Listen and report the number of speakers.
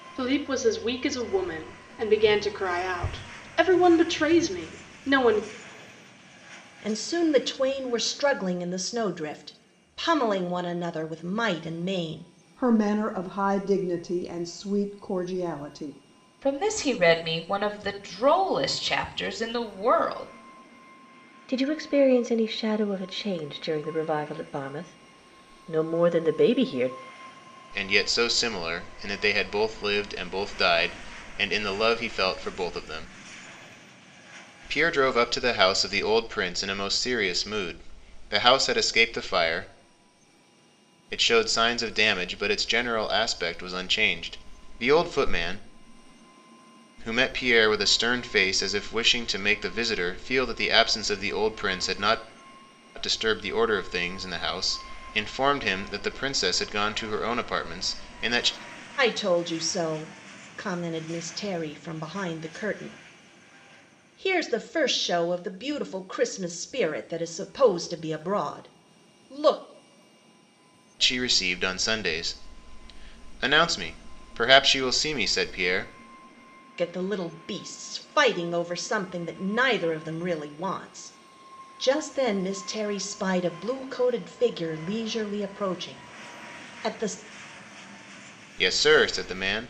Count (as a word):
six